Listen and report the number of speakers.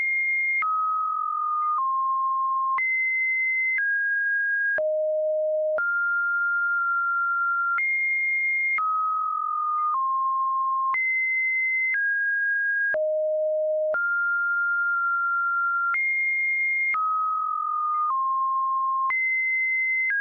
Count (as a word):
zero